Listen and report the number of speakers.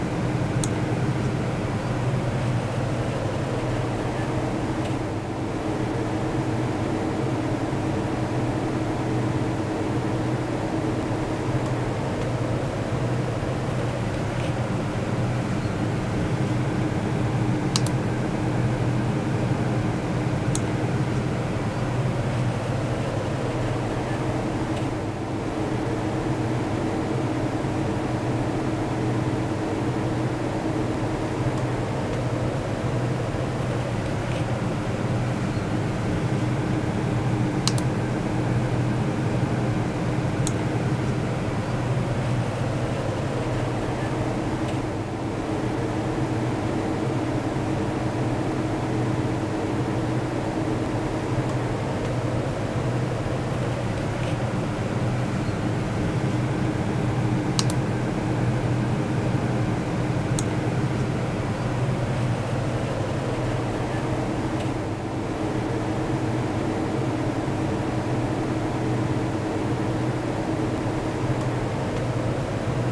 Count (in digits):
0